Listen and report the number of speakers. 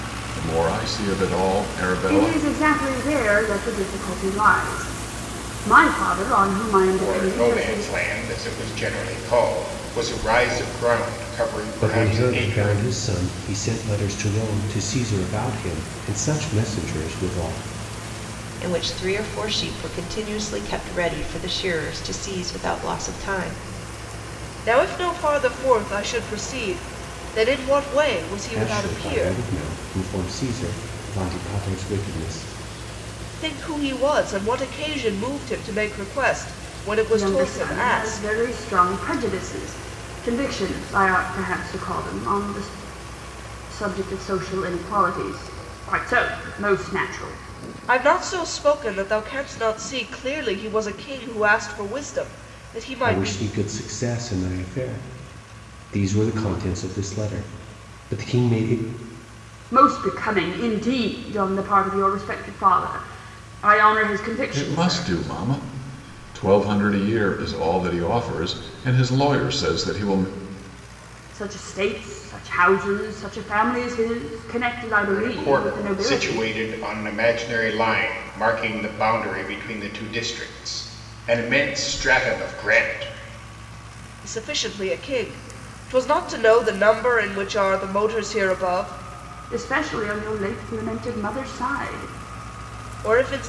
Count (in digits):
6